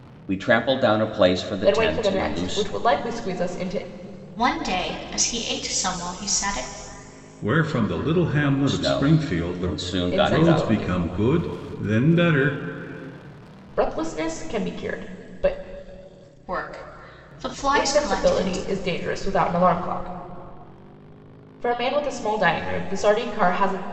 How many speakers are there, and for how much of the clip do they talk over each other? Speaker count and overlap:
4, about 16%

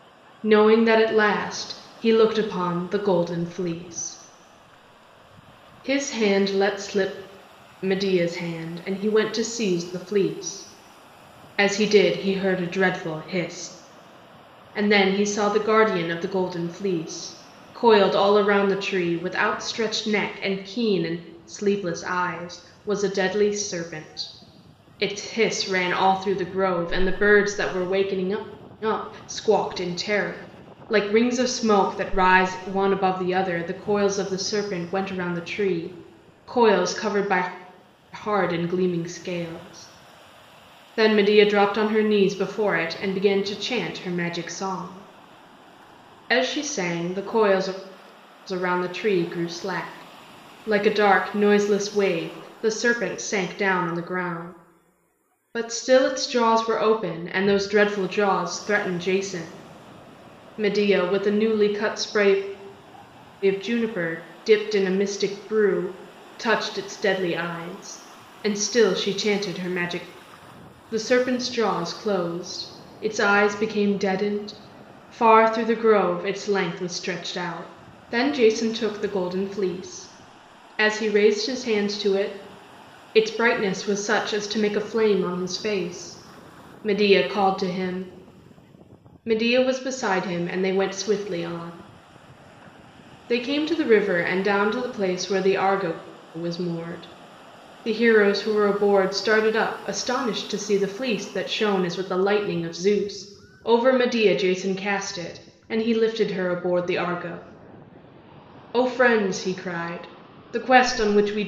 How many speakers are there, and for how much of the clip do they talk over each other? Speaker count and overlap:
1, no overlap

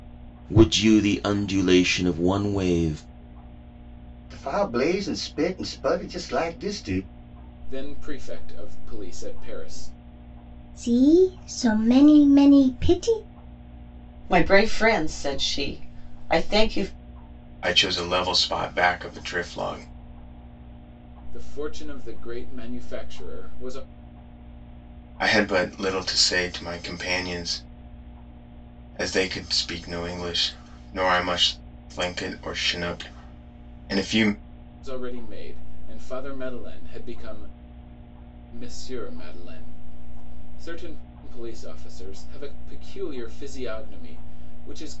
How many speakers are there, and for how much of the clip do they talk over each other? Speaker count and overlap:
6, no overlap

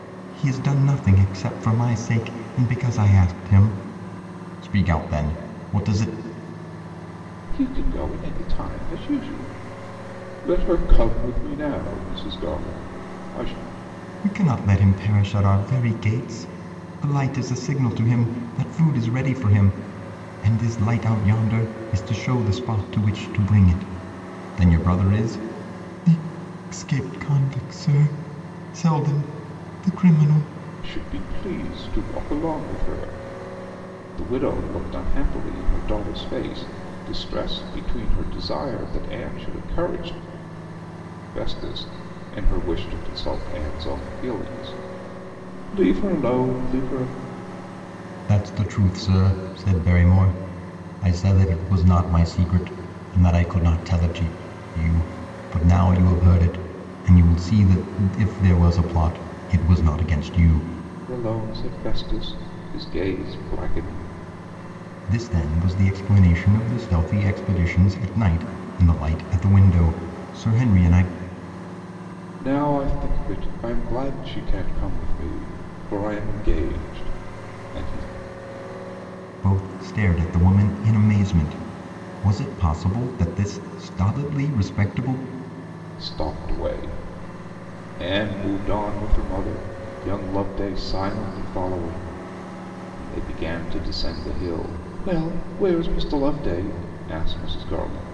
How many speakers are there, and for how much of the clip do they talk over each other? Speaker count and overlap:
2, no overlap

